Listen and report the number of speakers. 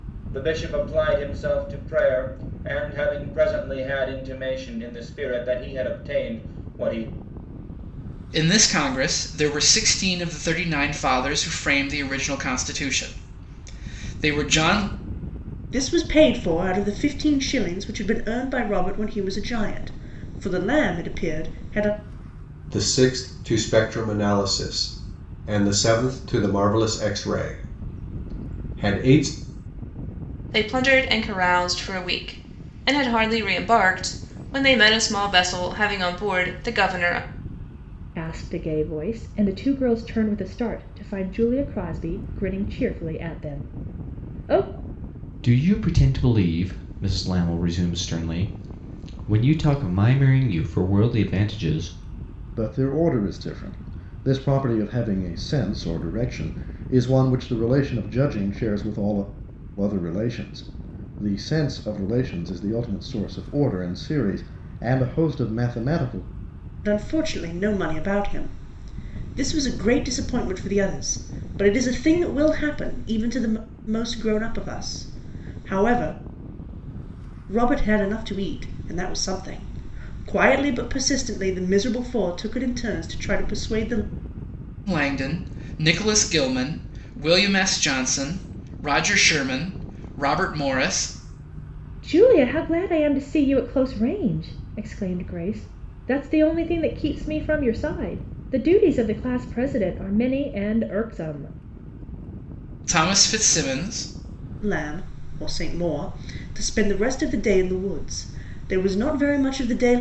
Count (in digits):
8